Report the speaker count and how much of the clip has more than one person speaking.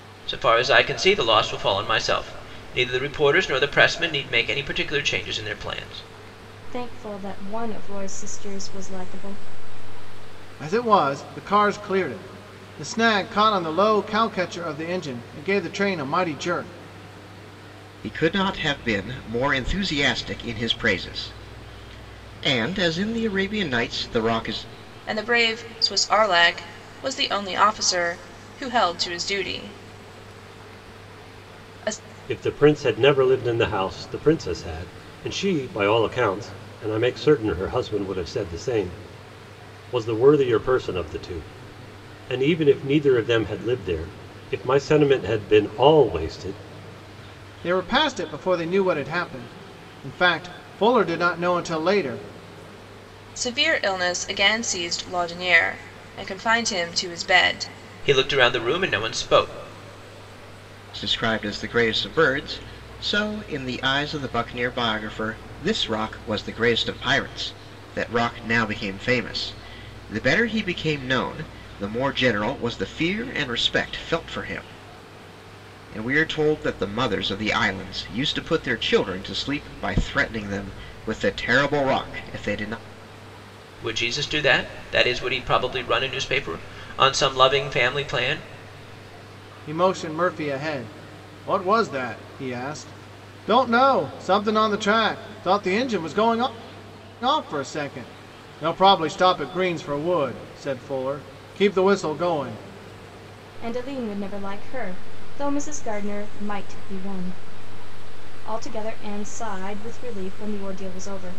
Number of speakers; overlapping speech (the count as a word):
six, no overlap